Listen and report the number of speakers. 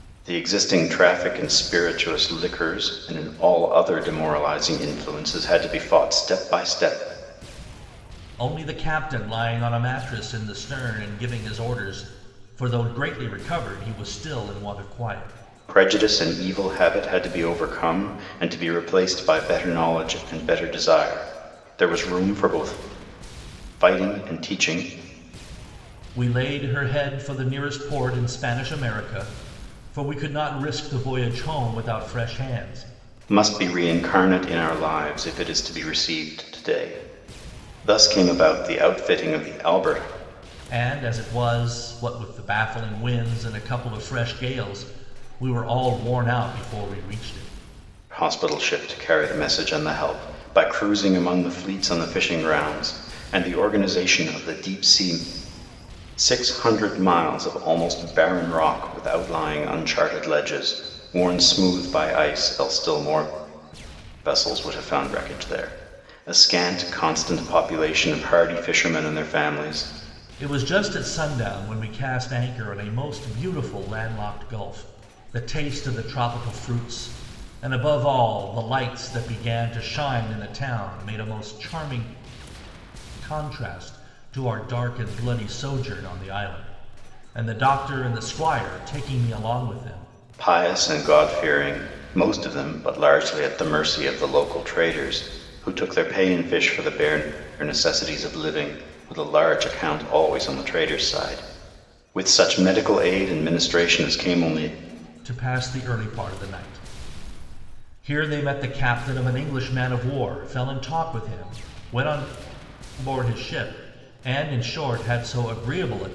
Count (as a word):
two